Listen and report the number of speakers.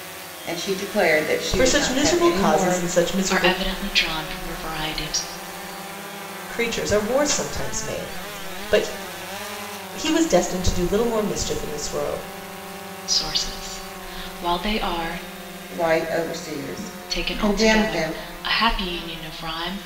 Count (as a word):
three